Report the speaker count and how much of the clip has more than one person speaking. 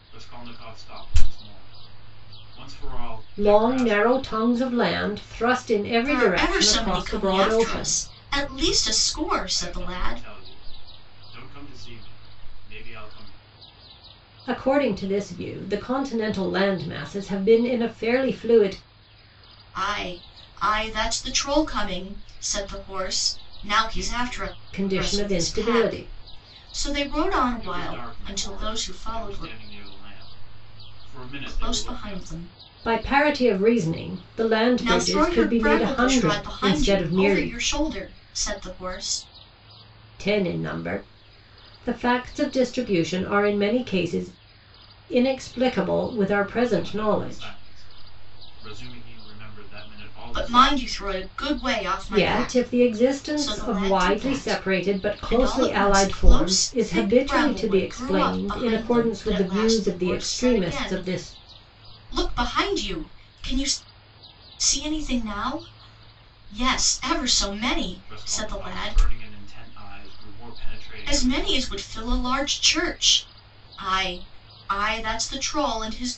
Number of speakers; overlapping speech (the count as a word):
three, about 33%